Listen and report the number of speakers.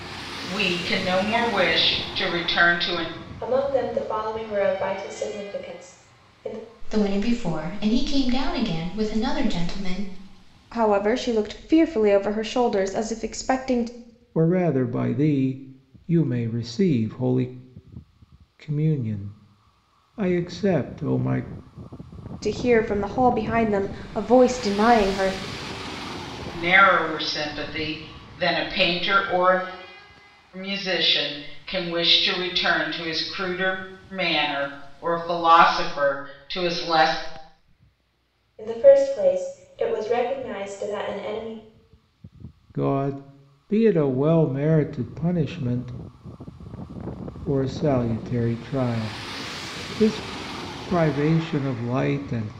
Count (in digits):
5